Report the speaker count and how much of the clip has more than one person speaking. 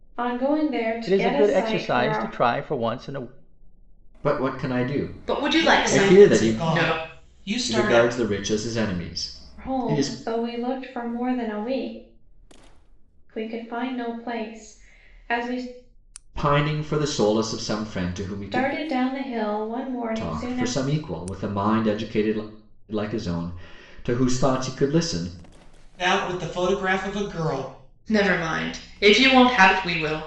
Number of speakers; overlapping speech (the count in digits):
5, about 16%